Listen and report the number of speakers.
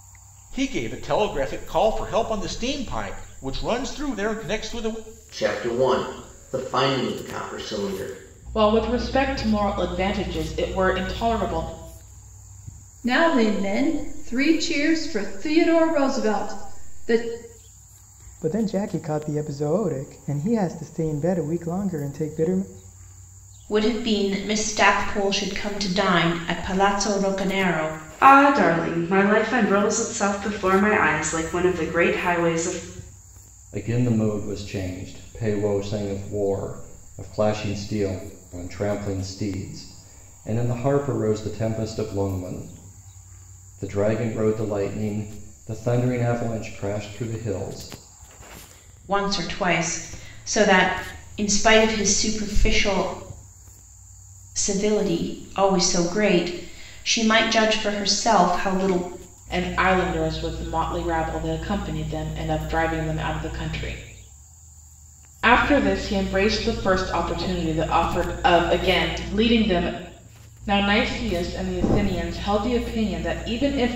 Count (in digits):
8